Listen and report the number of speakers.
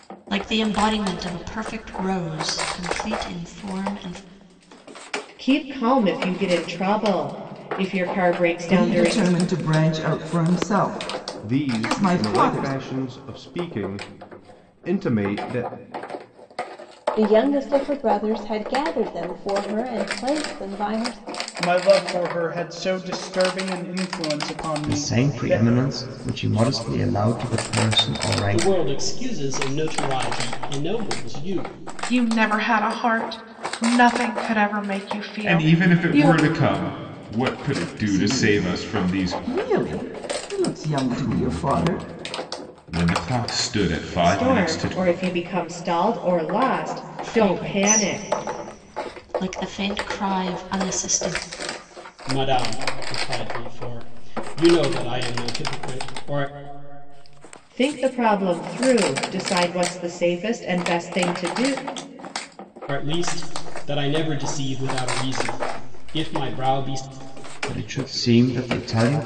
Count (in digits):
10